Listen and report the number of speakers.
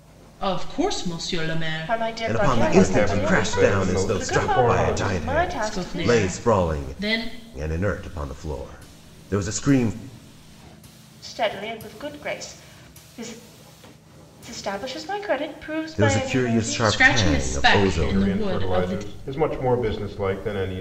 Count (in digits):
4